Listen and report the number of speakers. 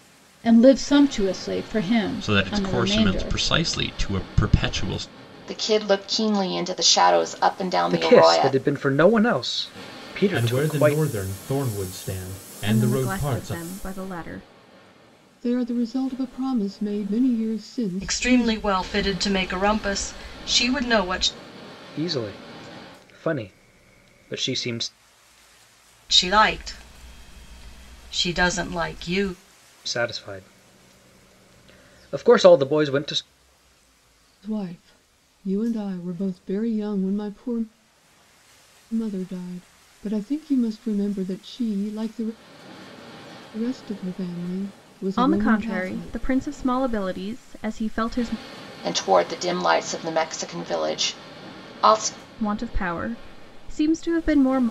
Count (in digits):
8